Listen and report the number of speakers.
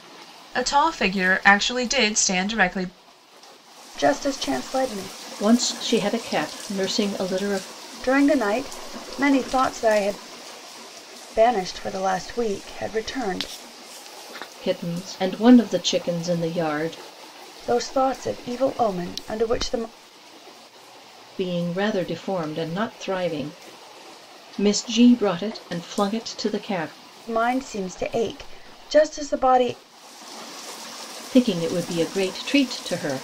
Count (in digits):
3